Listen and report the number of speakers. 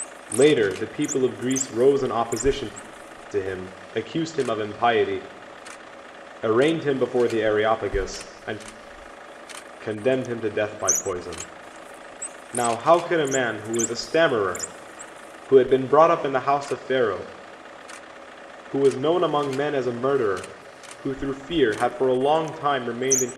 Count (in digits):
1